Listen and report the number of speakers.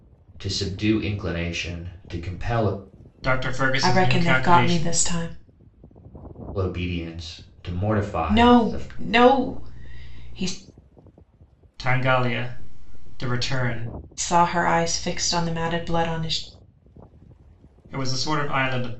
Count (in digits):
3